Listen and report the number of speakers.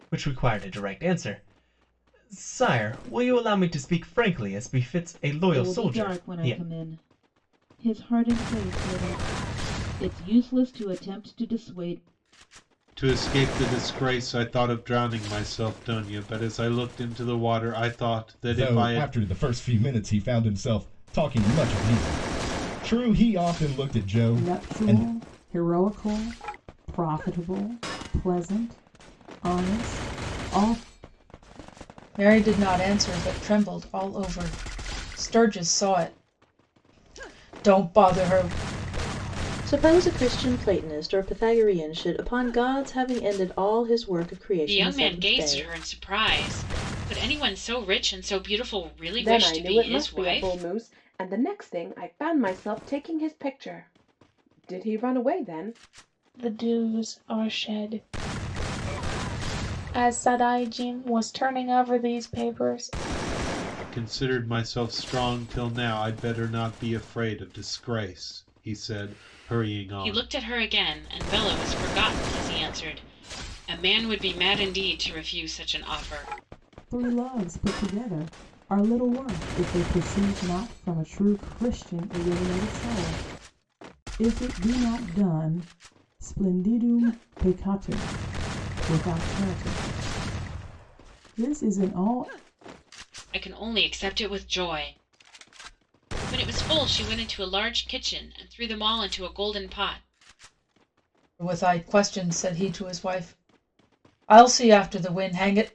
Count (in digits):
10